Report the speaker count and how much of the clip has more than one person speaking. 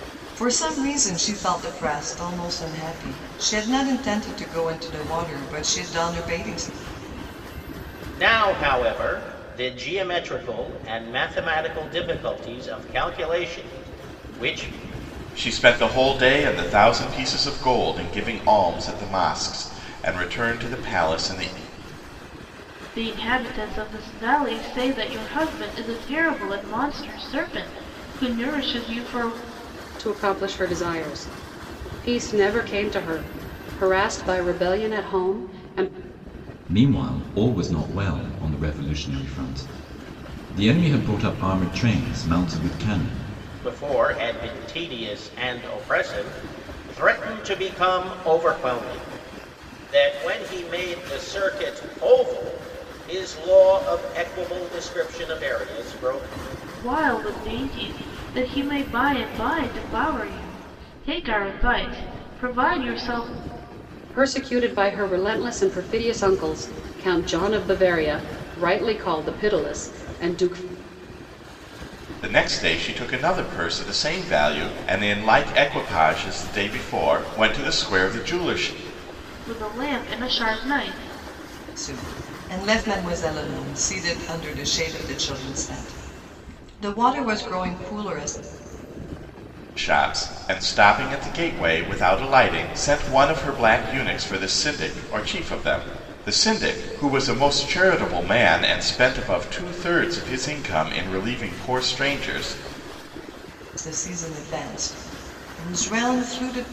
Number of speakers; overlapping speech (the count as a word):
six, no overlap